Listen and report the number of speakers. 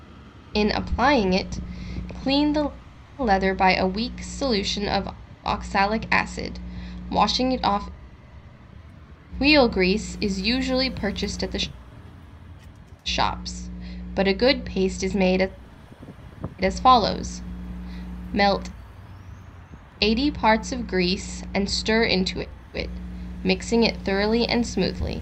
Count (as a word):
one